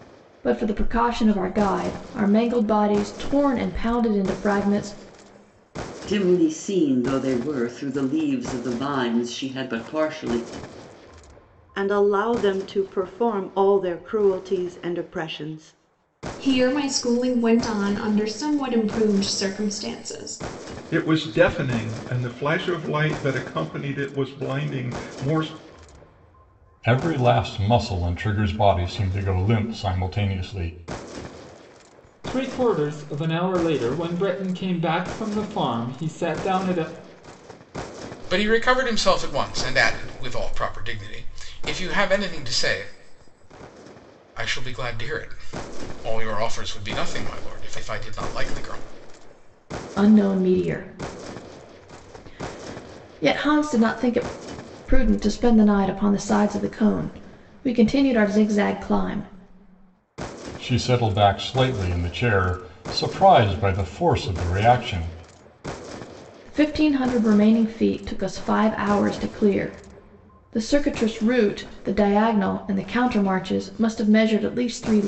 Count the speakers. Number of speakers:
8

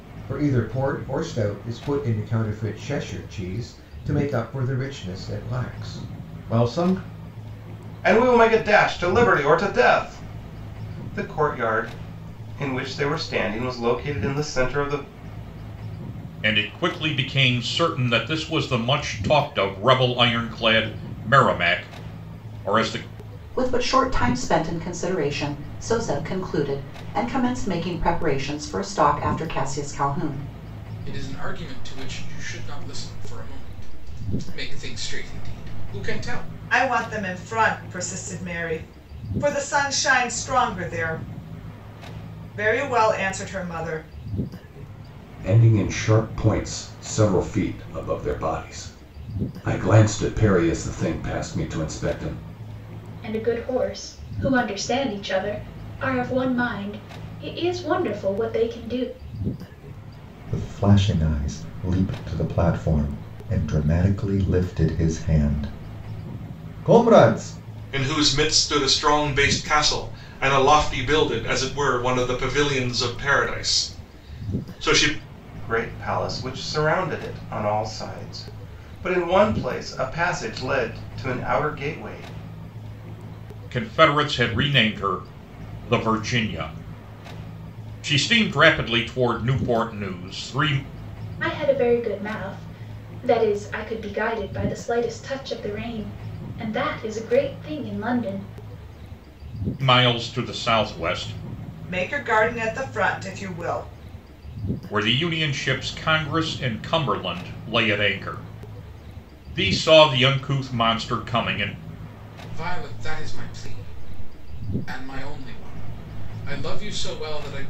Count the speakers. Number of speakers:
10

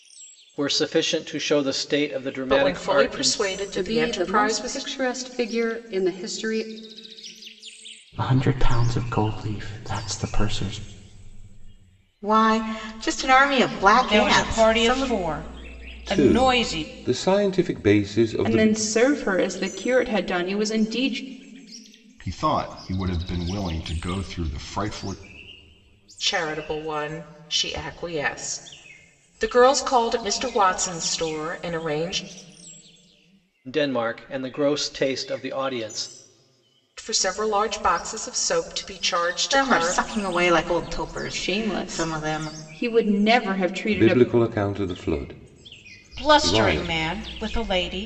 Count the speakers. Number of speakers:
9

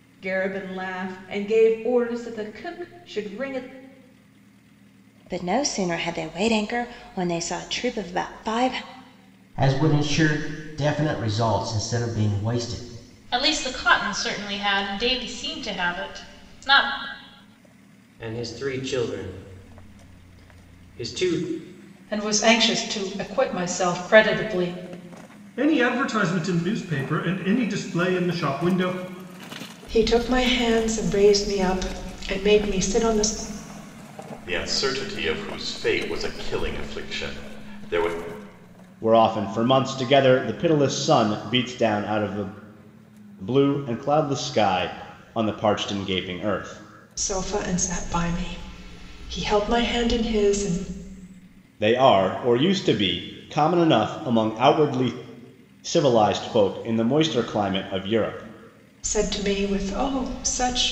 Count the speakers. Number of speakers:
10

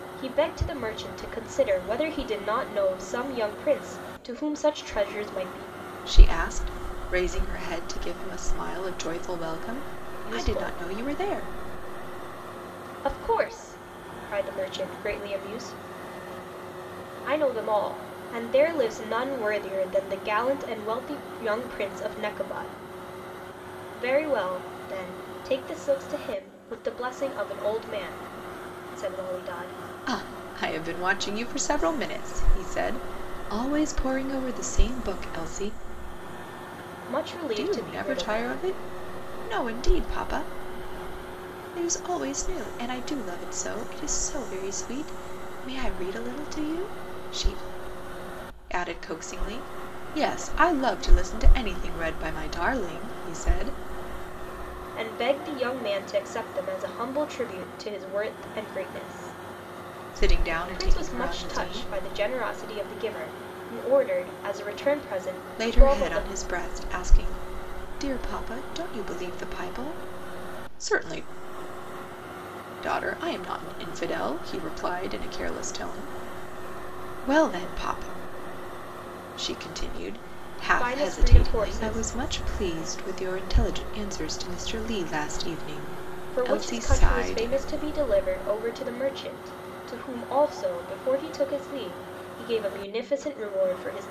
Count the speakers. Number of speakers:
2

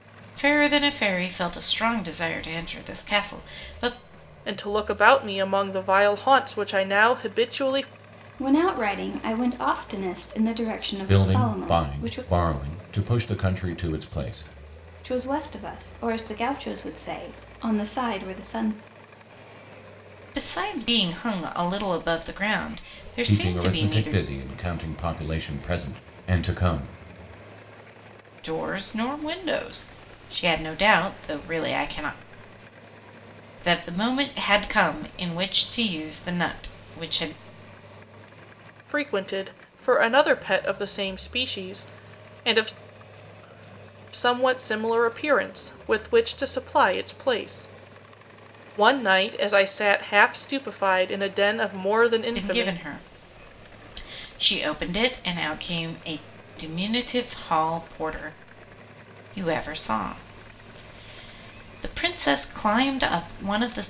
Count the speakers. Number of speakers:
4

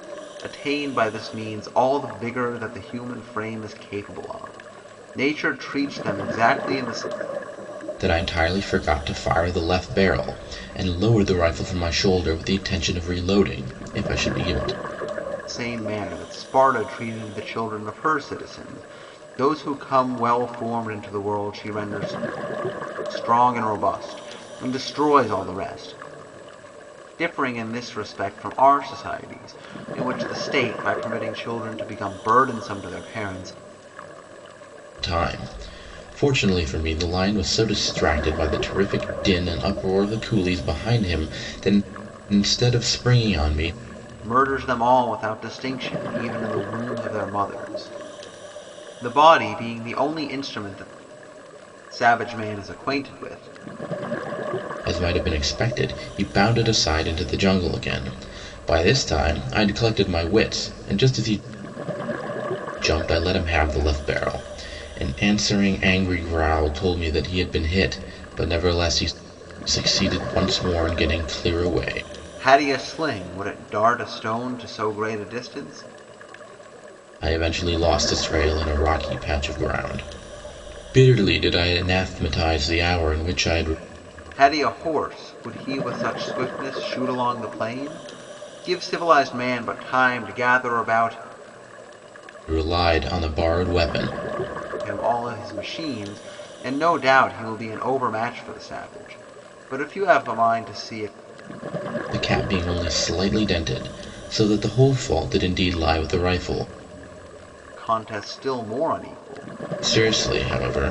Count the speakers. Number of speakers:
2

